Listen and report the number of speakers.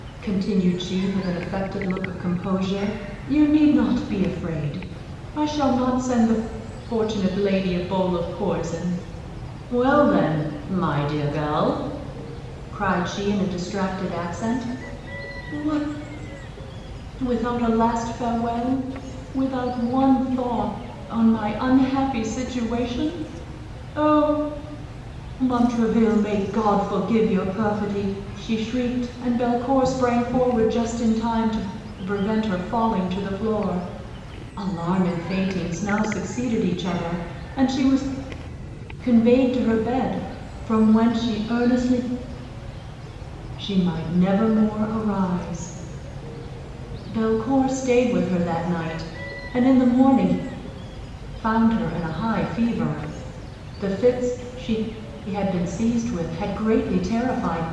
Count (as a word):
one